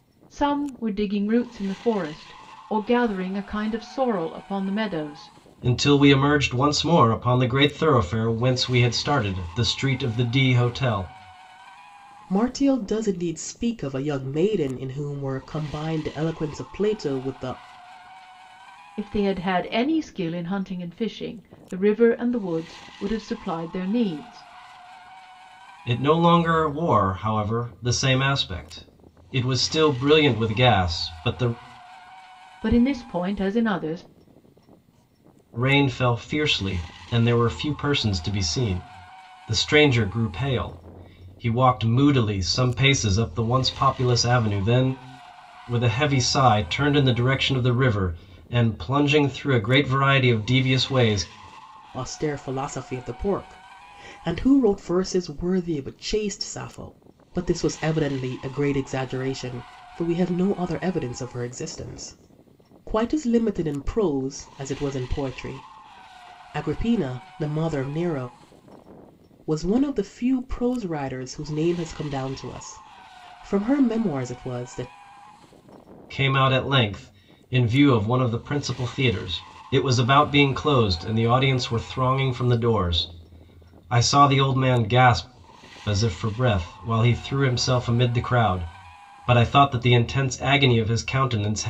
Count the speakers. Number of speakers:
3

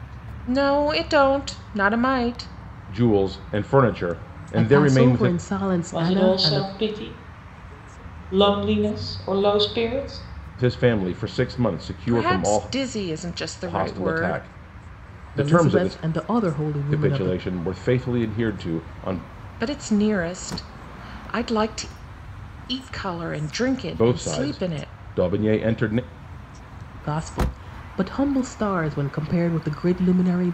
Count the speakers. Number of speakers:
4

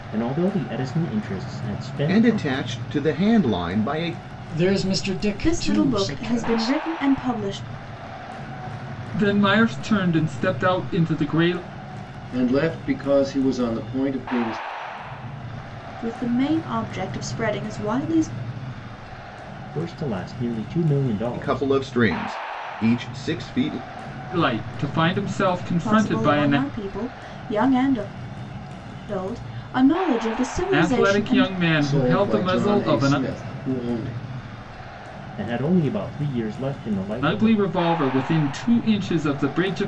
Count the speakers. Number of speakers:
6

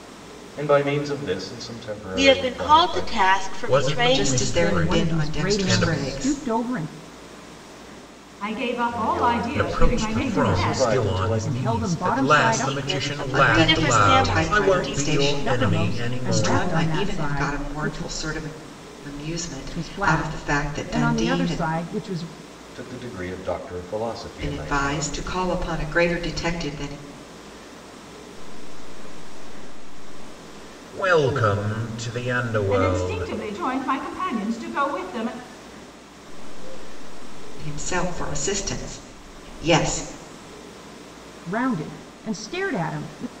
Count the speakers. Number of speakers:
7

